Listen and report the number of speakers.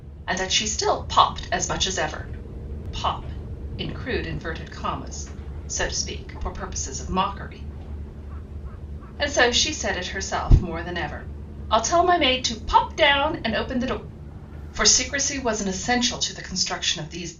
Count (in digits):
1